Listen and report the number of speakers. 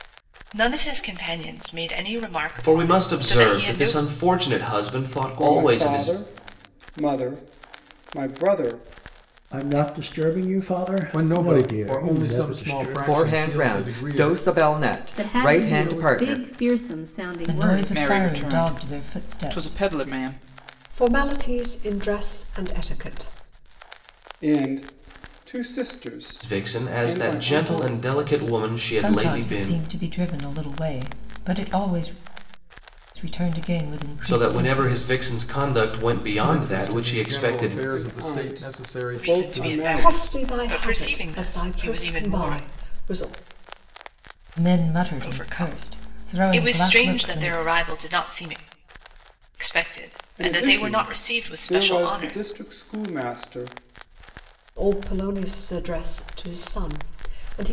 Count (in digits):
10